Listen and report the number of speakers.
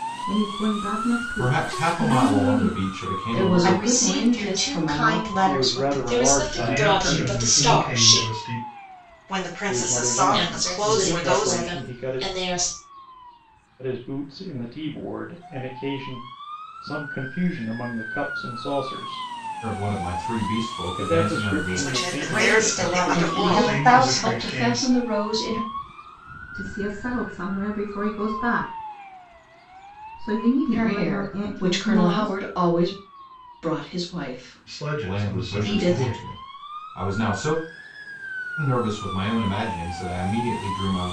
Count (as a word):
eight